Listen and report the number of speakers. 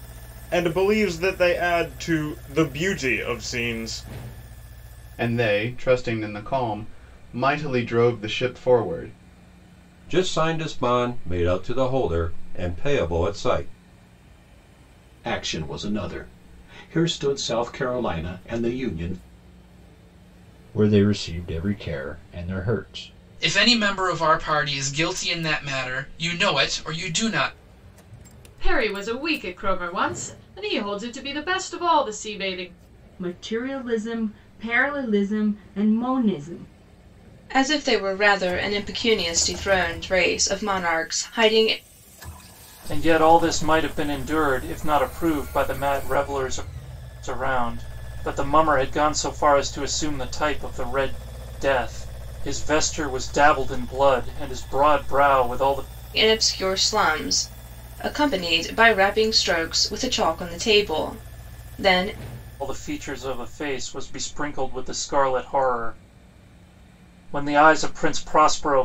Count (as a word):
ten